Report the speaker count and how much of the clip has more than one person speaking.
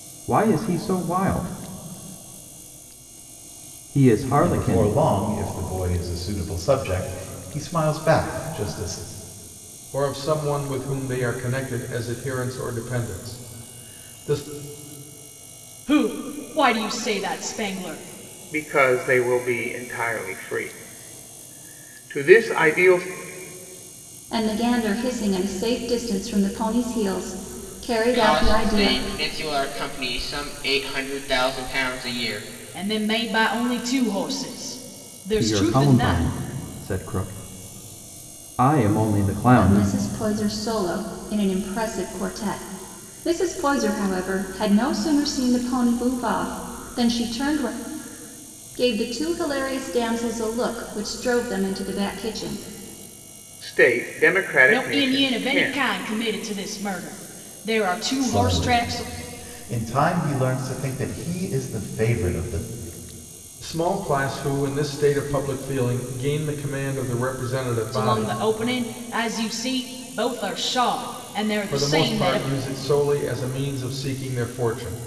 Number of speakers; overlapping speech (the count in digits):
7, about 8%